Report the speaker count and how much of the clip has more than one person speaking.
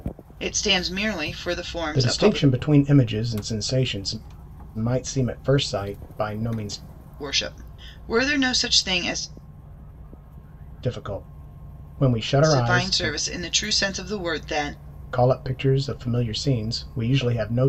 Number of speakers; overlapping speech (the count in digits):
2, about 8%